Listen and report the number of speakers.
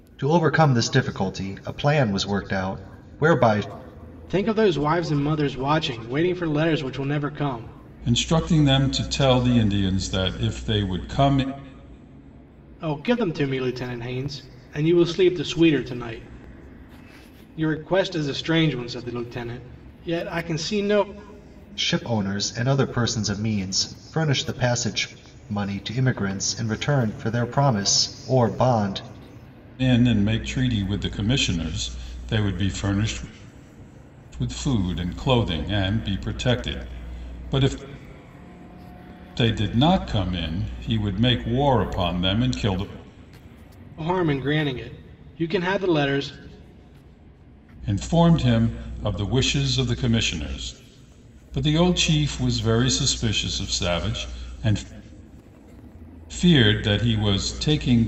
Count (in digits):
3